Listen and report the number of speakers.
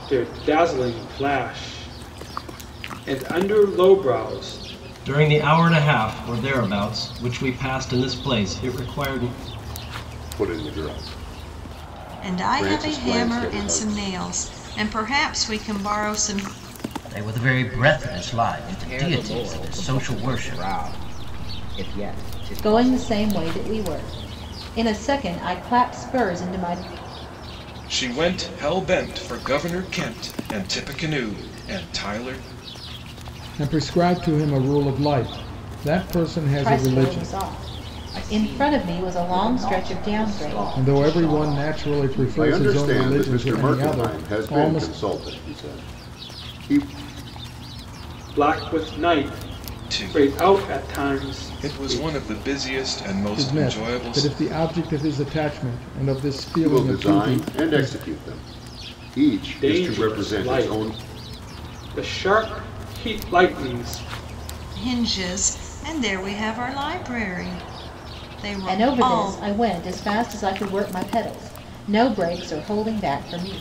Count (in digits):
9